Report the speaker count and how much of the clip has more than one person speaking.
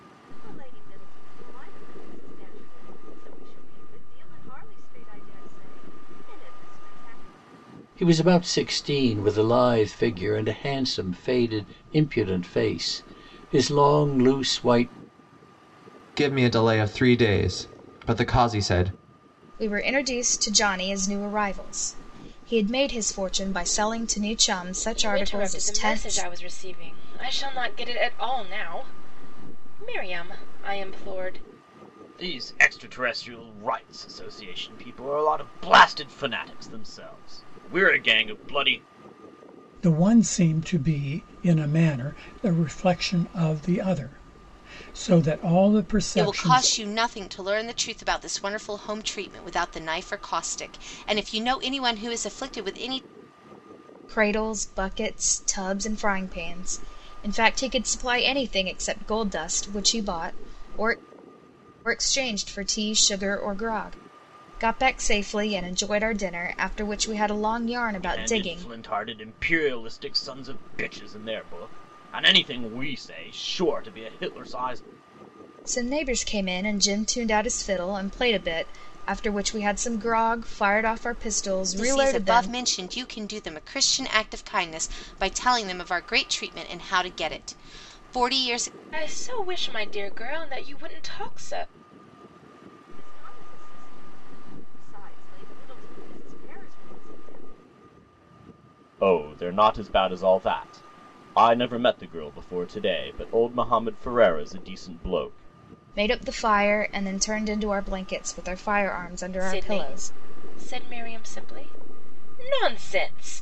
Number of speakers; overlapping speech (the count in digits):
8, about 4%